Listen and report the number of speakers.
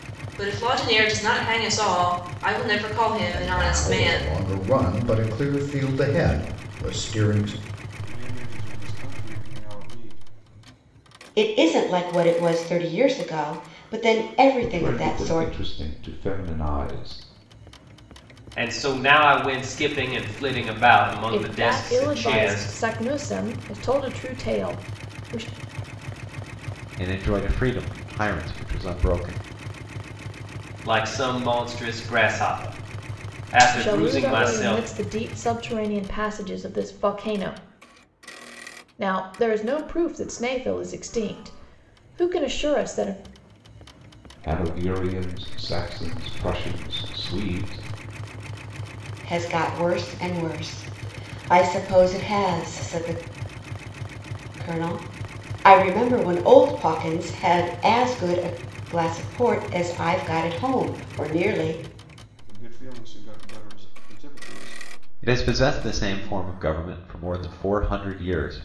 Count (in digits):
8